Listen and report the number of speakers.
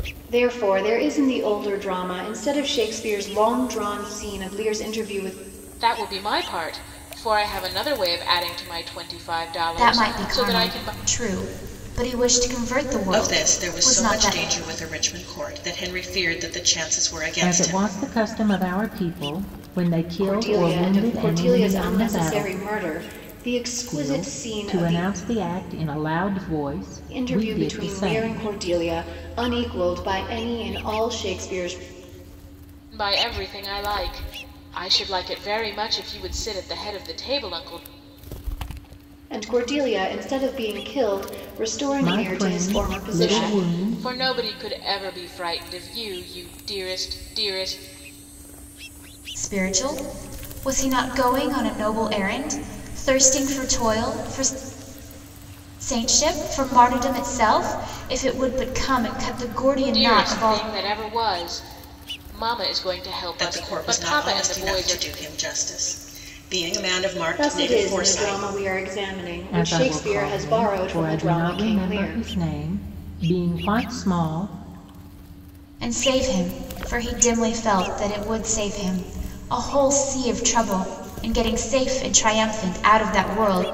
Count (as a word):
five